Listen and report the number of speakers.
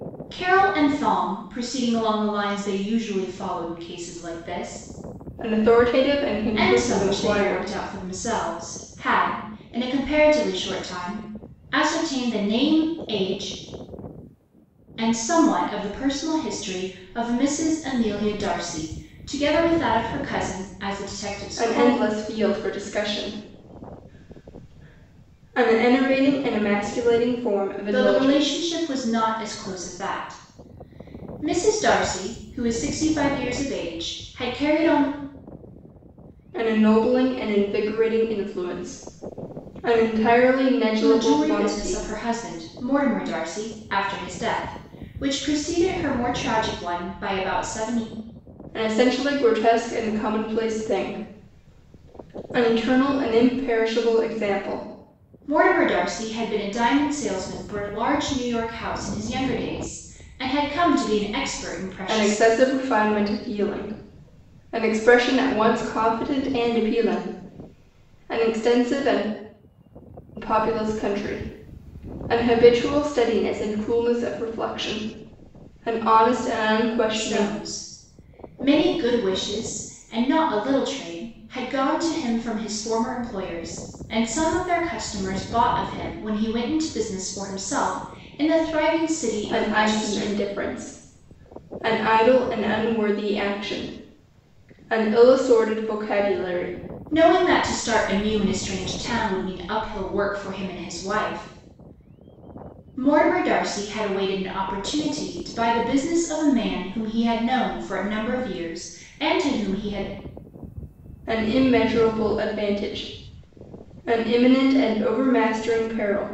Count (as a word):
two